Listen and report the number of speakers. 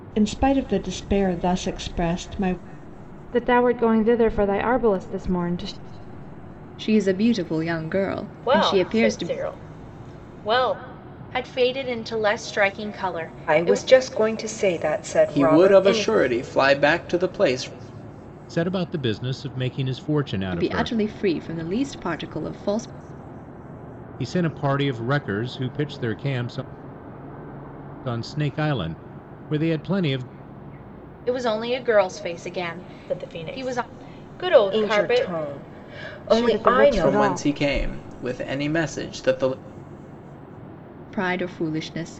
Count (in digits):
8